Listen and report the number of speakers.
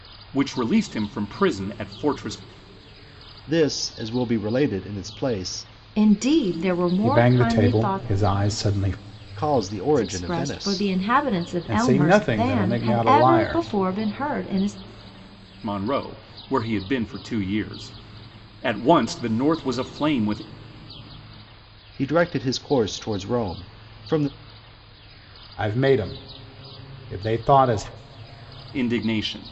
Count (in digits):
4